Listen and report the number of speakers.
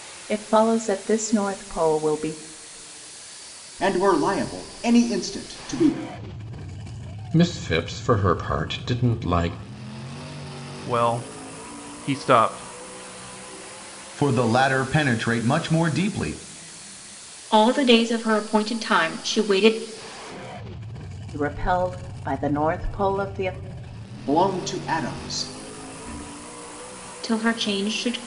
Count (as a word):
six